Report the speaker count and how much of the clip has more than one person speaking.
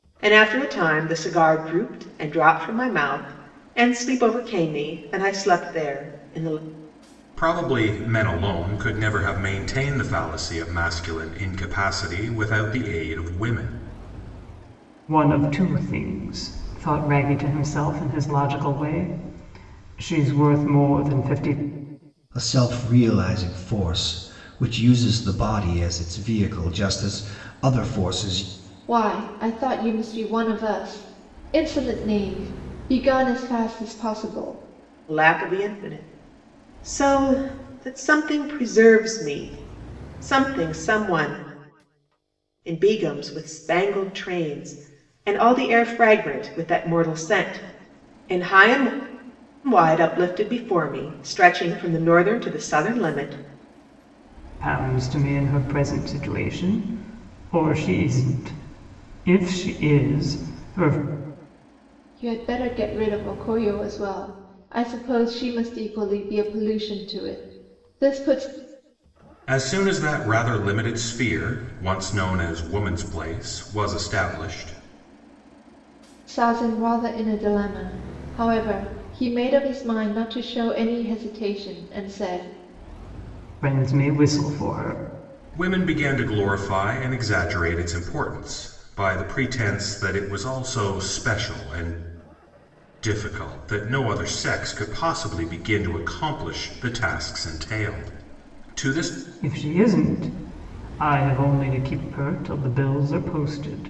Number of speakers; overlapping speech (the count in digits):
5, no overlap